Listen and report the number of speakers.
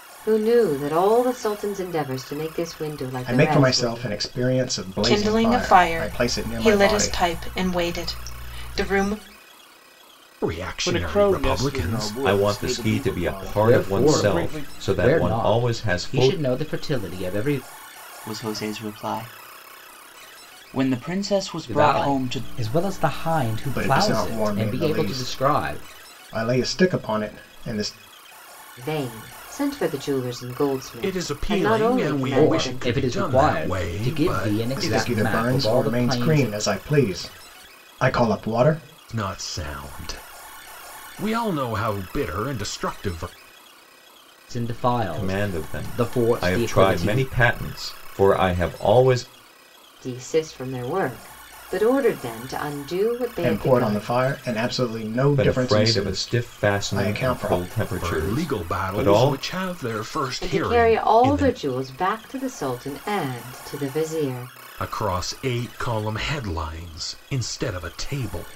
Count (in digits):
8